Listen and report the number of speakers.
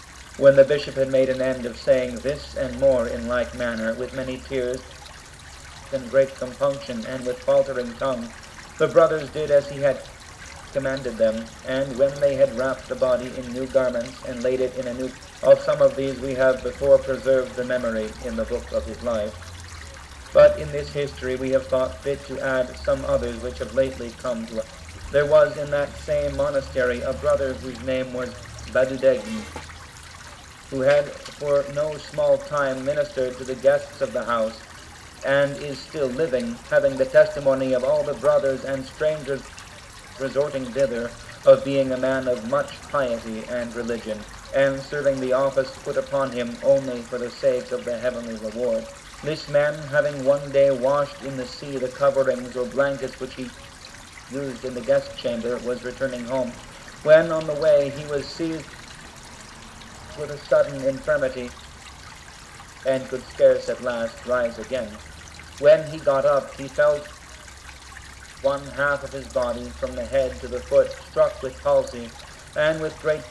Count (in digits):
1